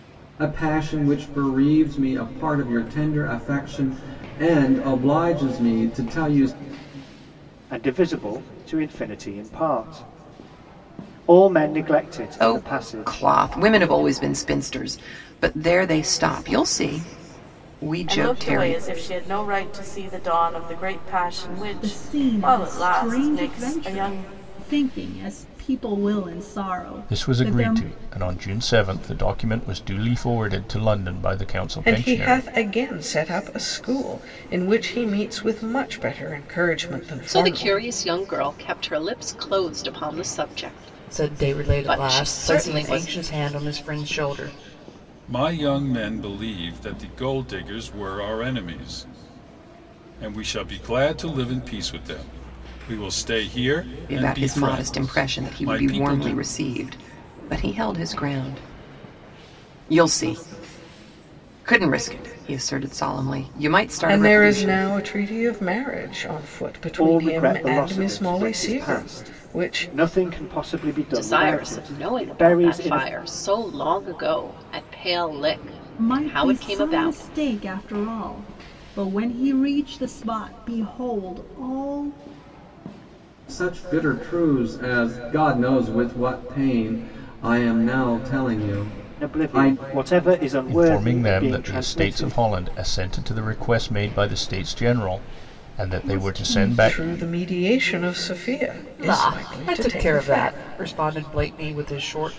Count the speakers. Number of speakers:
ten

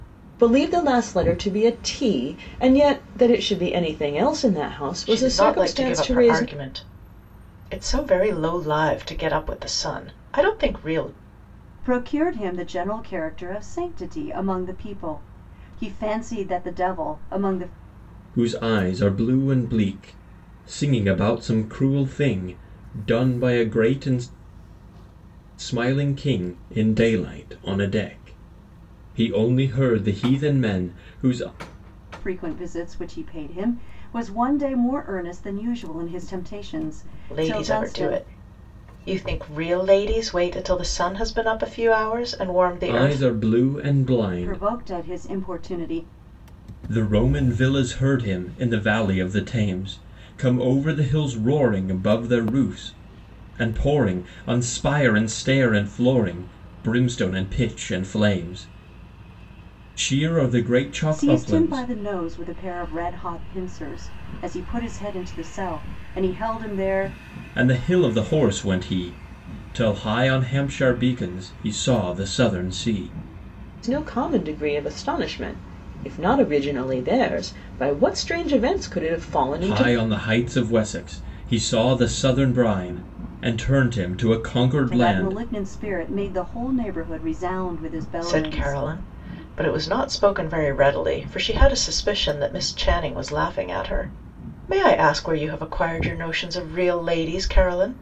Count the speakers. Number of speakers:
four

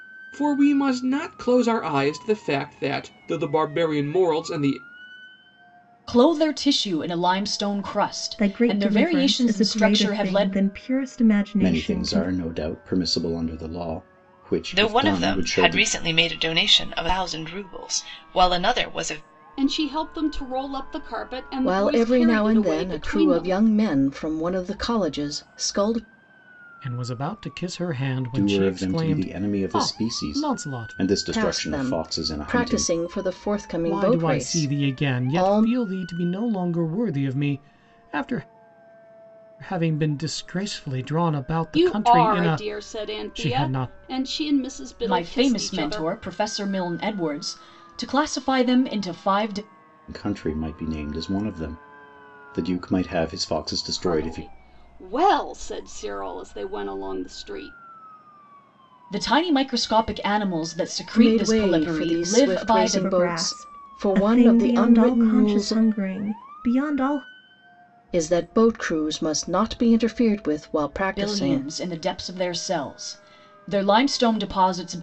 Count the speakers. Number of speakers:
eight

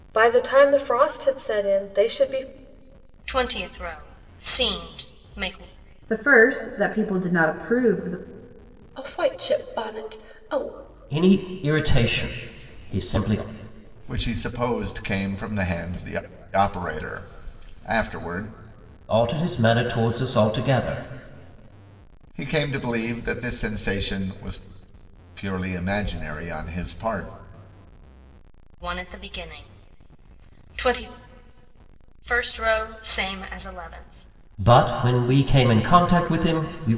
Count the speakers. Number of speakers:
six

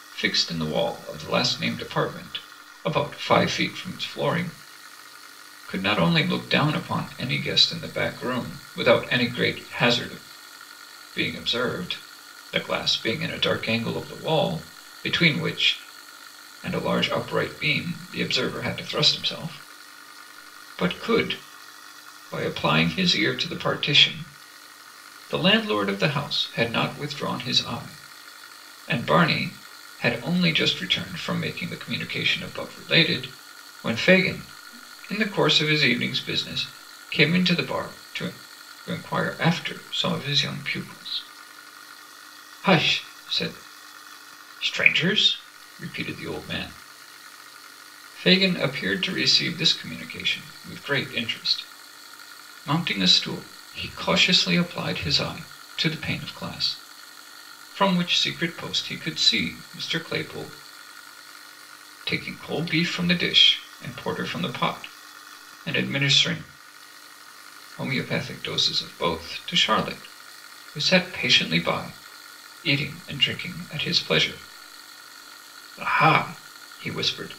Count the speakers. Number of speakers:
one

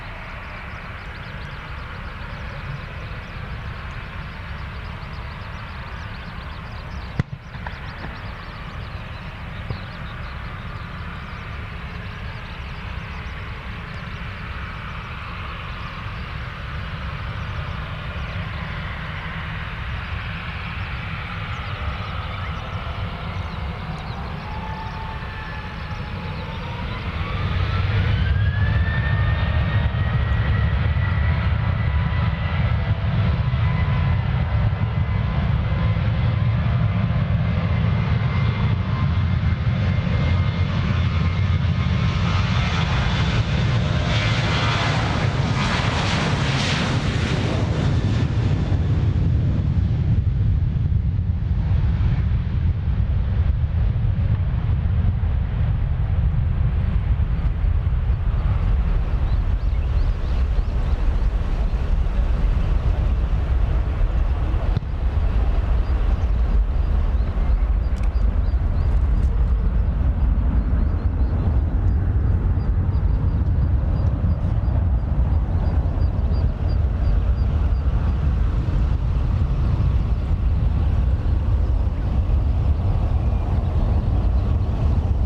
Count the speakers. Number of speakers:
zero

